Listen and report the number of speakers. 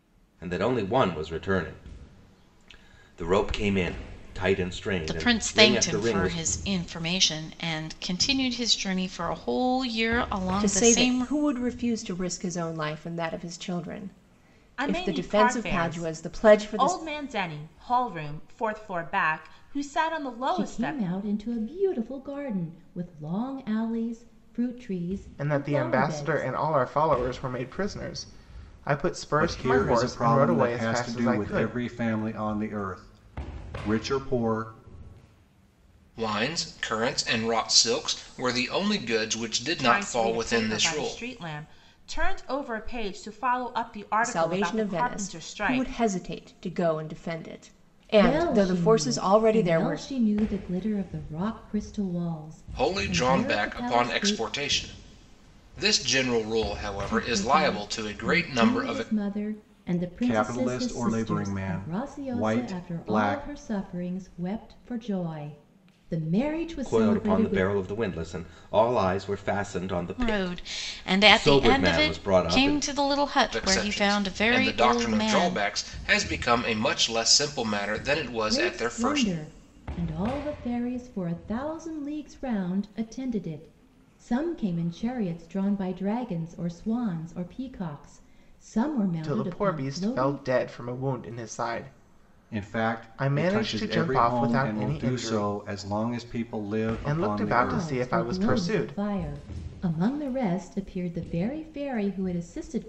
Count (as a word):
eight